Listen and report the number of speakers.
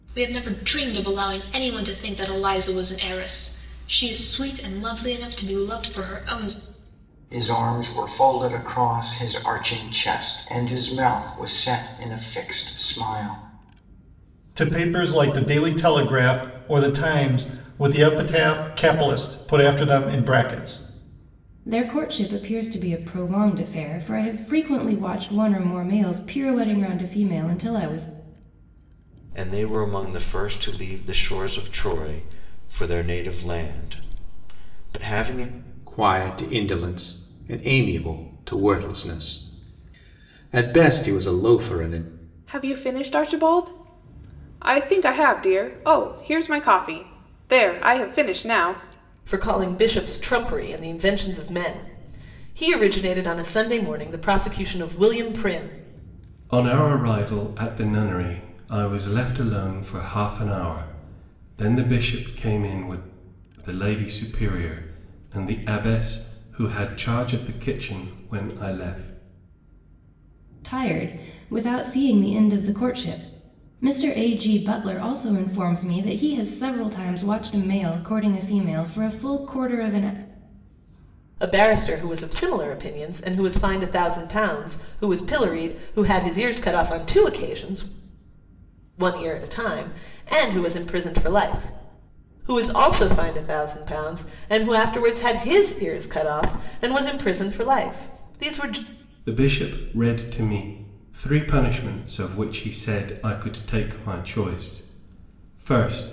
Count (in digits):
9